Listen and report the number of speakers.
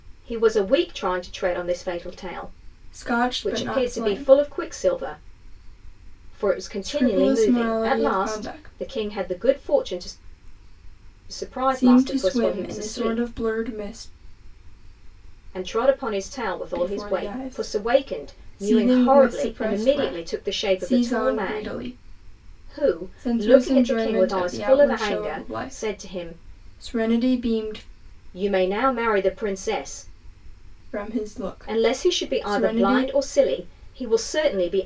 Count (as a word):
two